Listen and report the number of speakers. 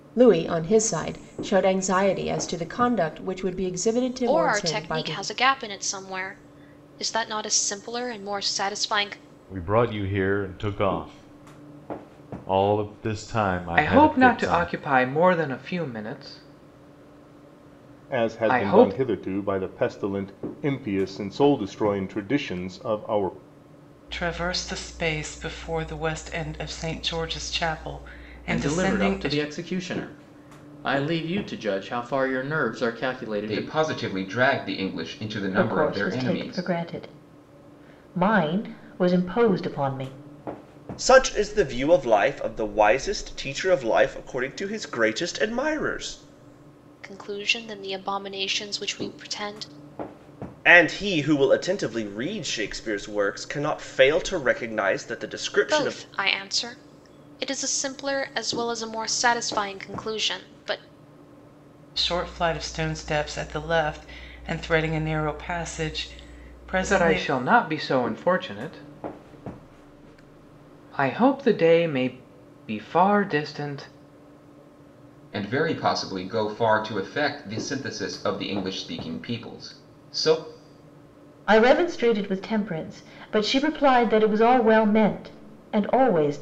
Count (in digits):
10